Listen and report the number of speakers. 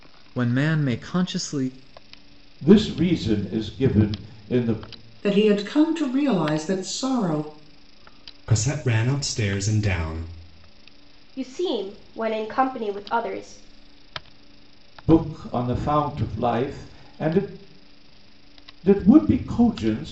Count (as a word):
five